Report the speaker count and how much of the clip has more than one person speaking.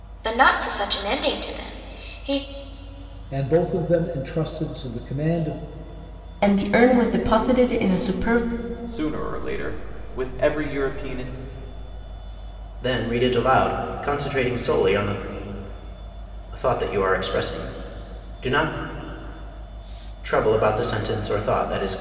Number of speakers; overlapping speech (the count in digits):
5, no overlap